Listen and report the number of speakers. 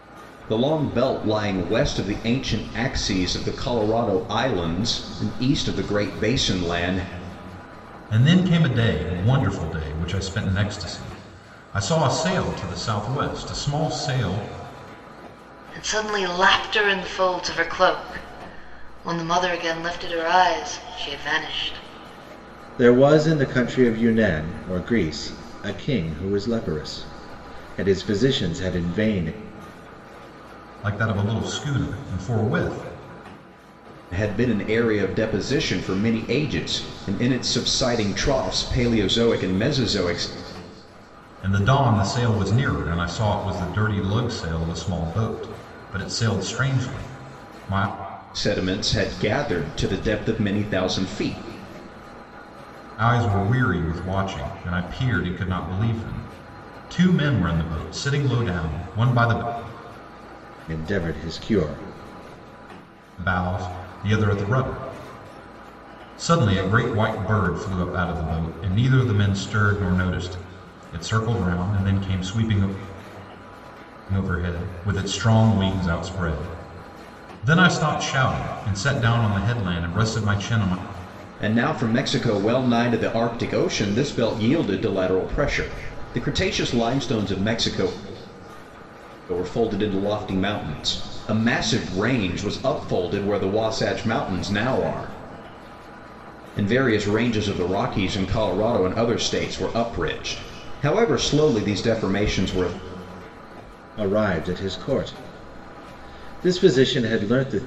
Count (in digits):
4